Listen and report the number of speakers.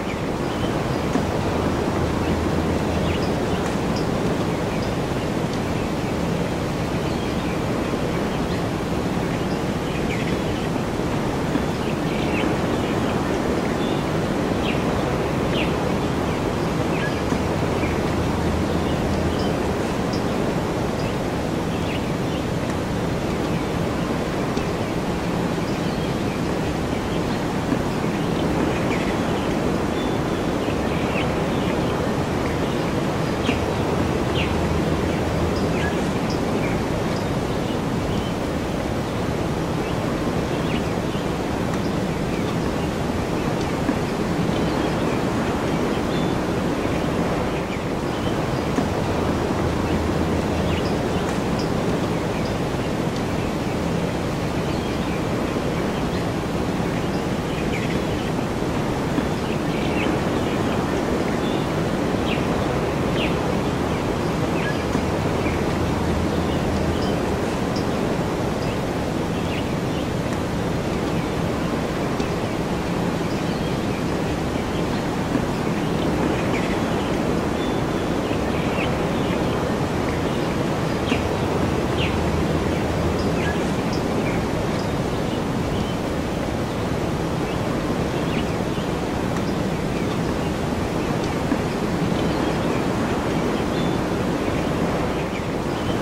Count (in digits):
0